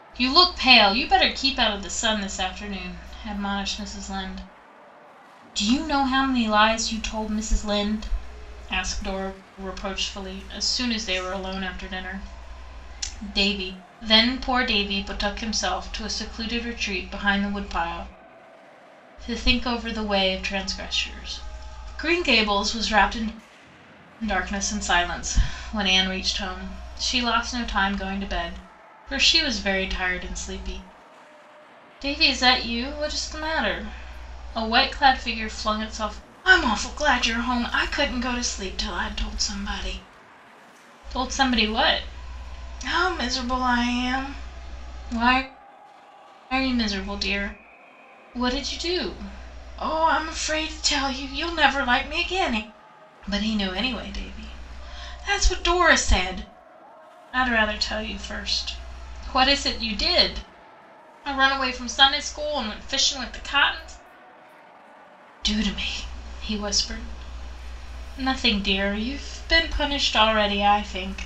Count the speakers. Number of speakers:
1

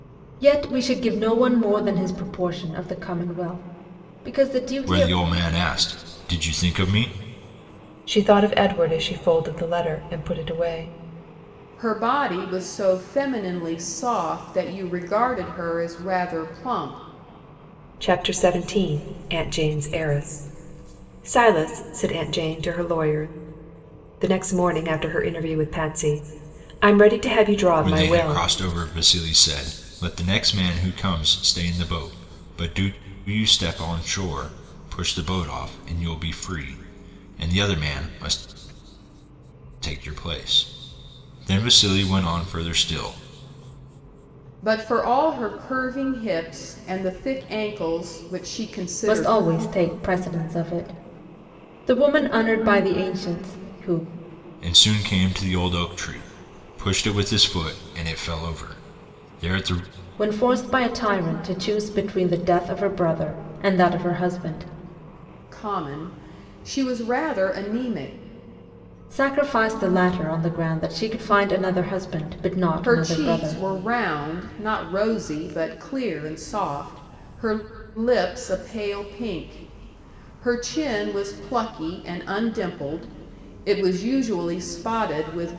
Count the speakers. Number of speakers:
4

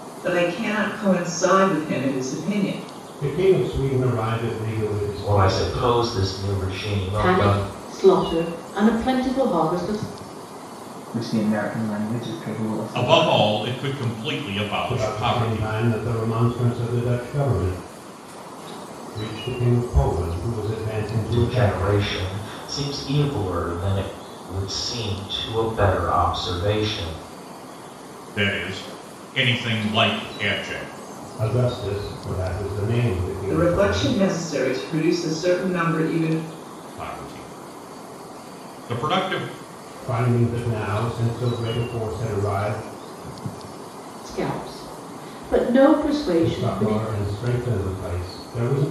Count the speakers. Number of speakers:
6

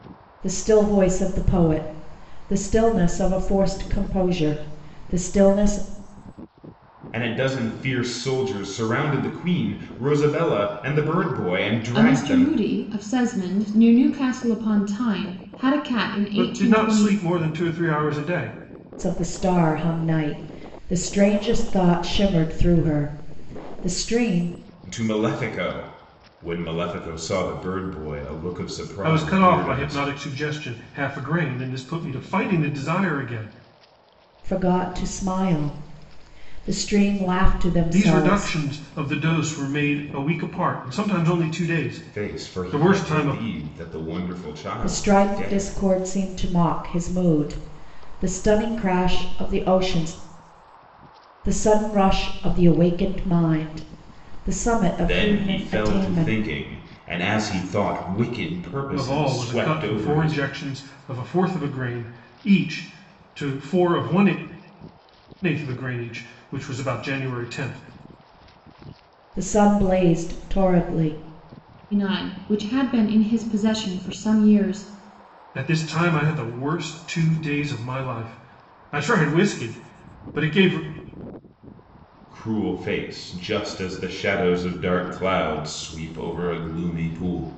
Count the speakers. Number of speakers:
4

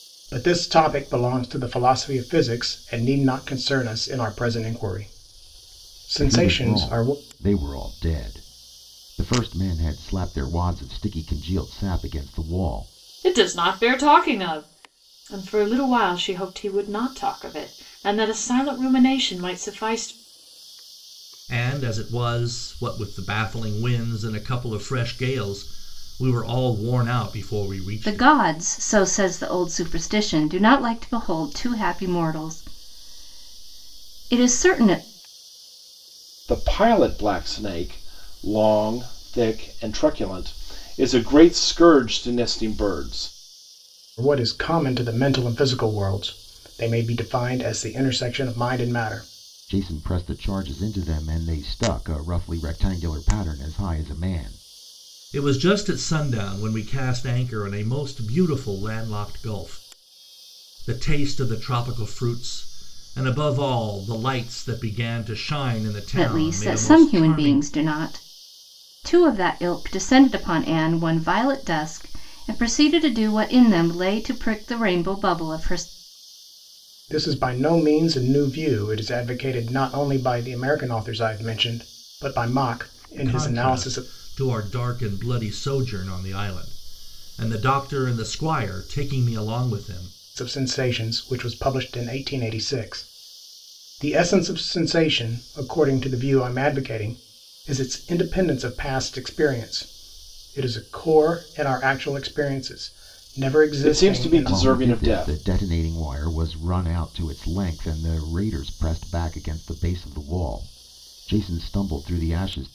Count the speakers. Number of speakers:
6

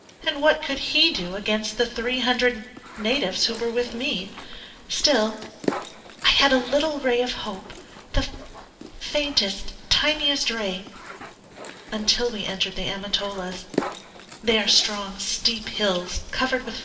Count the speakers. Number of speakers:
1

